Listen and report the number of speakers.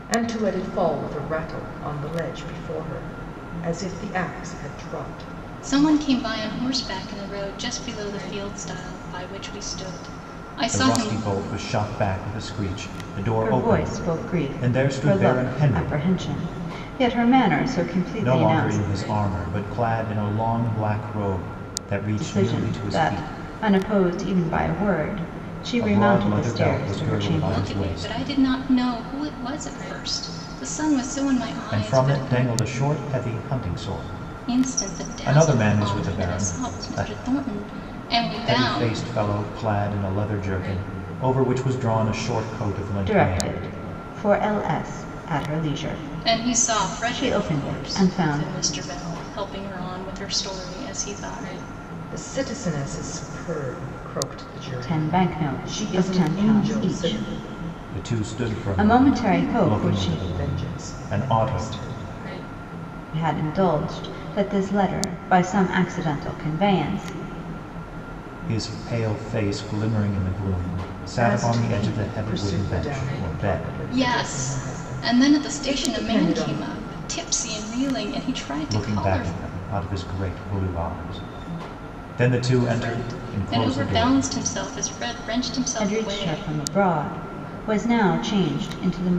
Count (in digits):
4